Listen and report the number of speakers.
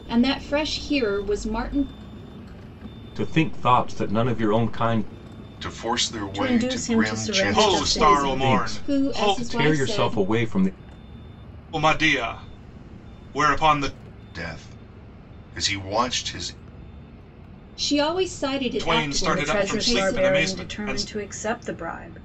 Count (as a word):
five